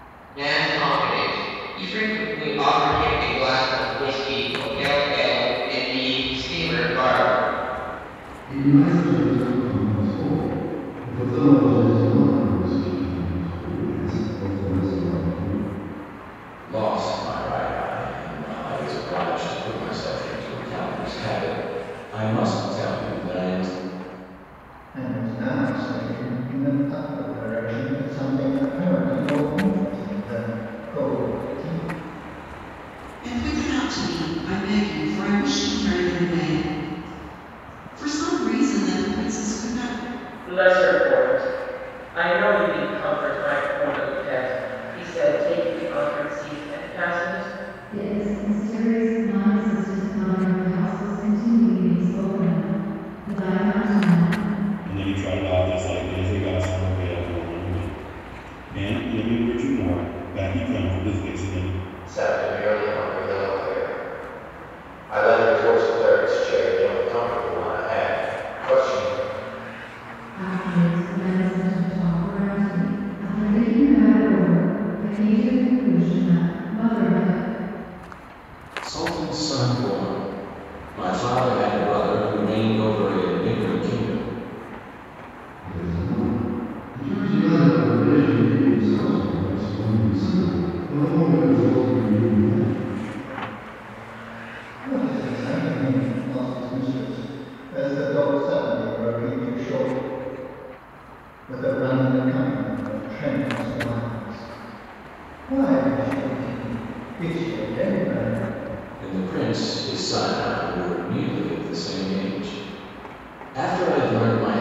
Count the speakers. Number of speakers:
nine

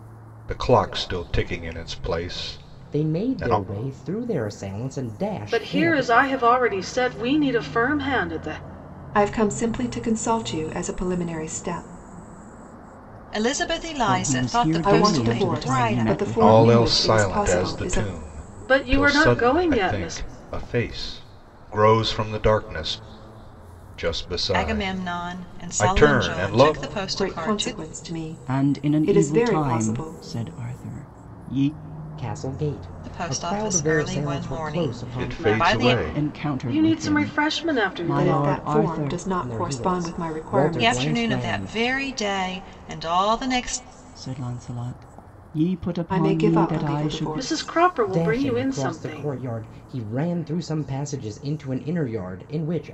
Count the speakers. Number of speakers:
six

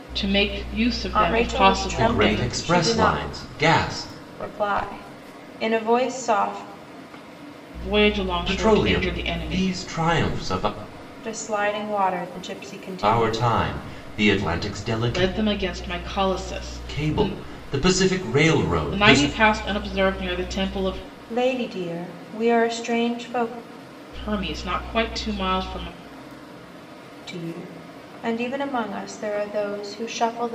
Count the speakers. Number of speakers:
three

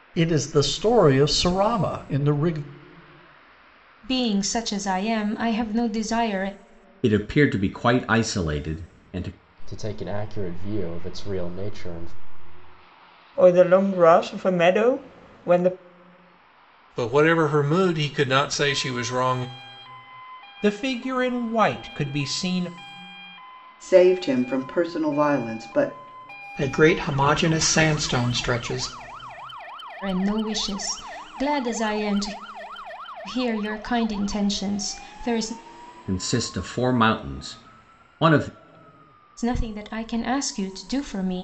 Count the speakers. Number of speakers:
nine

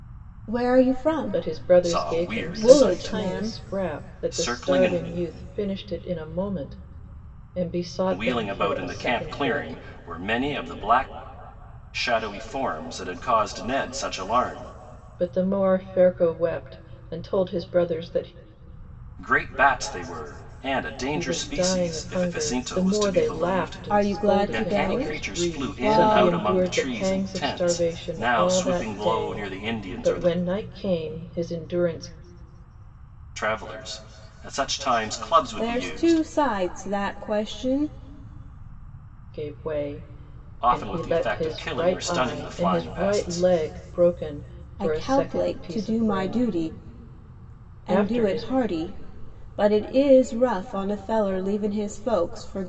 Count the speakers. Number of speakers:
three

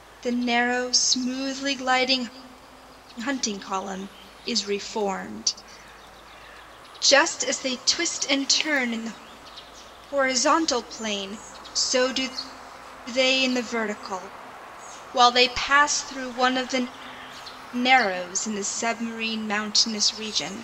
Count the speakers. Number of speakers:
one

